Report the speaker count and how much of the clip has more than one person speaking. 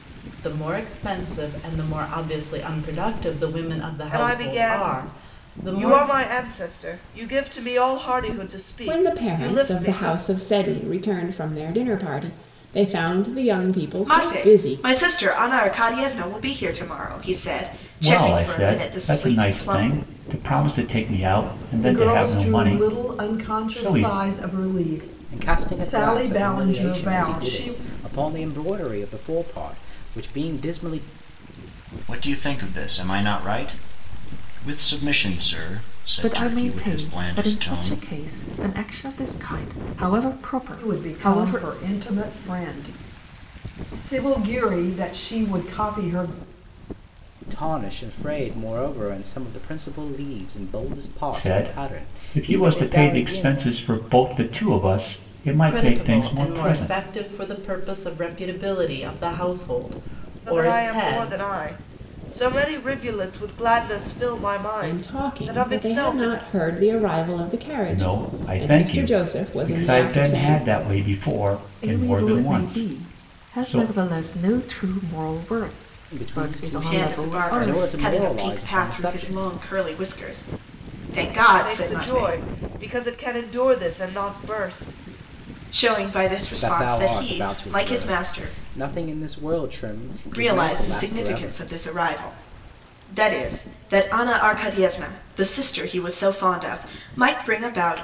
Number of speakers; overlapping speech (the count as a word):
nine, about 33%